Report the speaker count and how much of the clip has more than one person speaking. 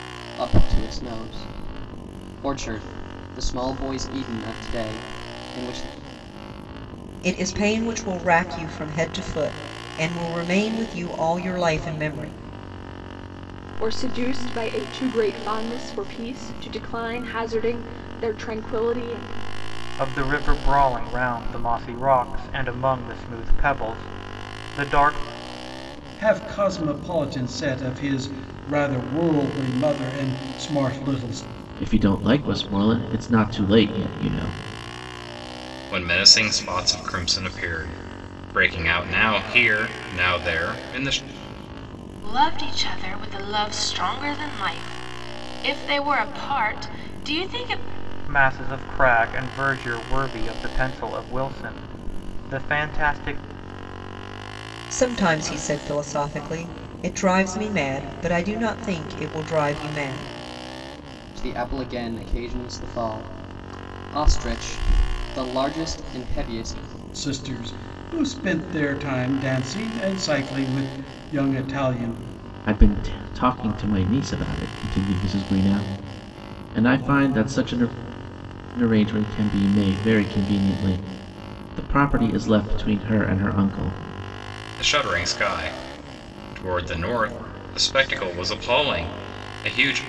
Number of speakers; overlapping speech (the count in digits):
8, no overlap